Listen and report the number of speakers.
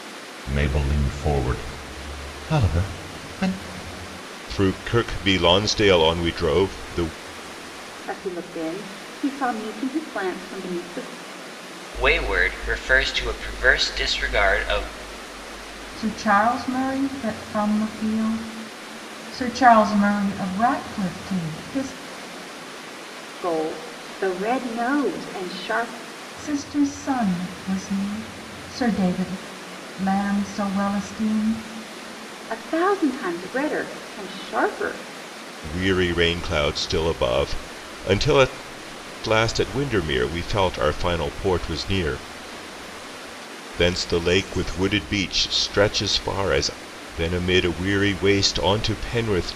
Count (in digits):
5